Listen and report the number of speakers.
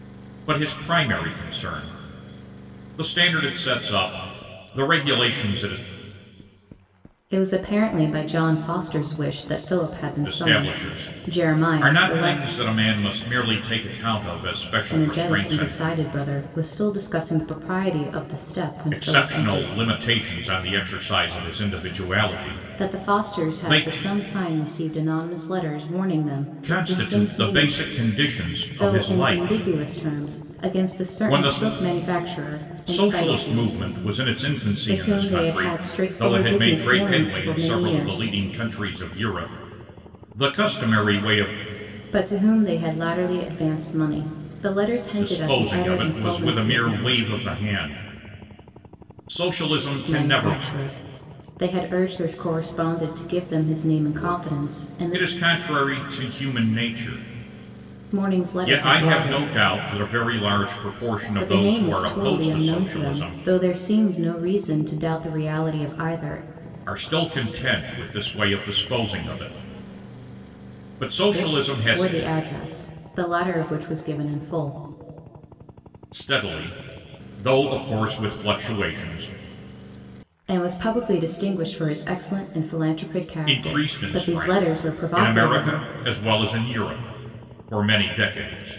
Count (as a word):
two